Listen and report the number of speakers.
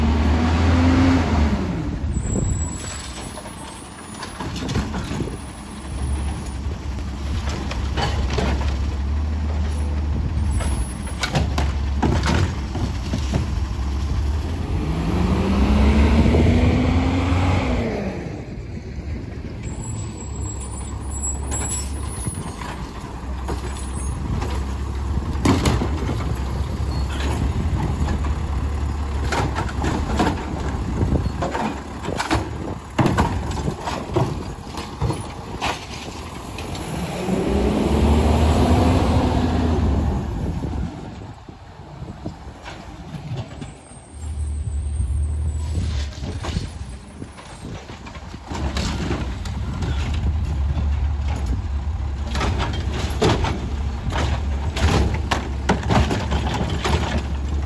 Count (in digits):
0